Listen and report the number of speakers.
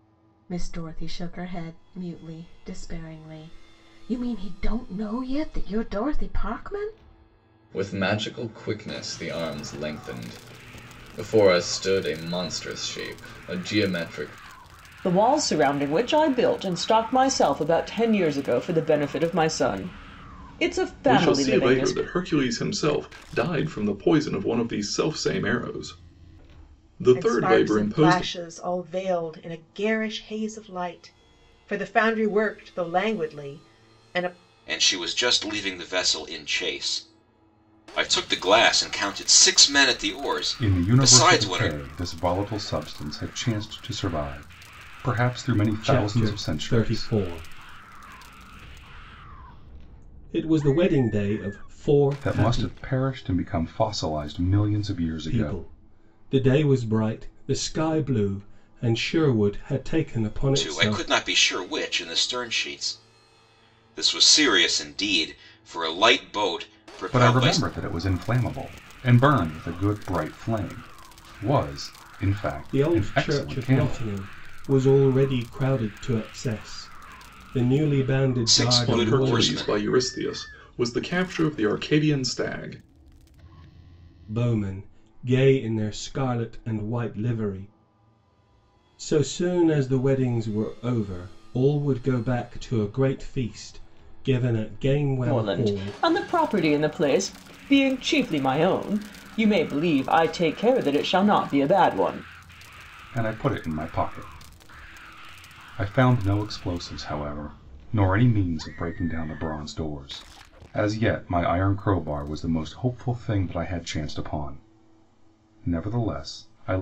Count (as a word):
eight